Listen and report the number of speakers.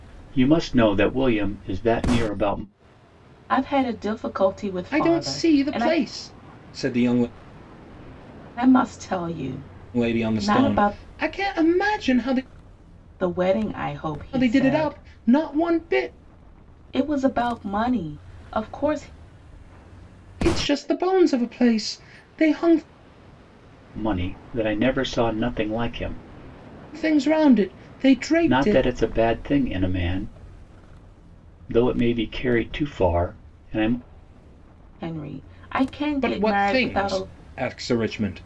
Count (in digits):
3